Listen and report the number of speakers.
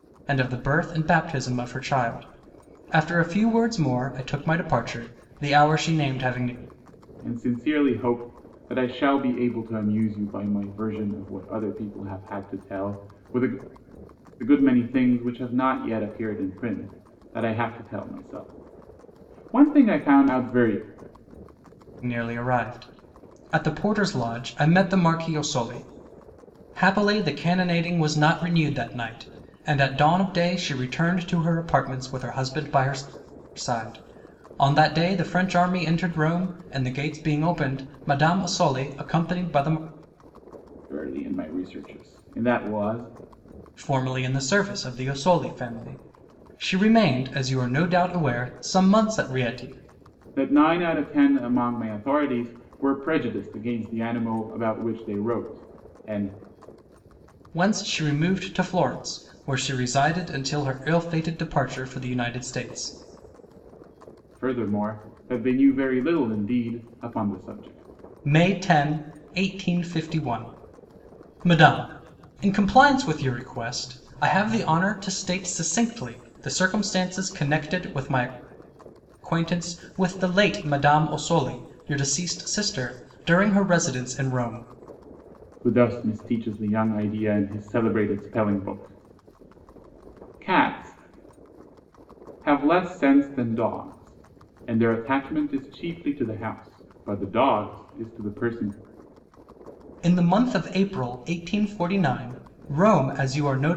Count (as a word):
two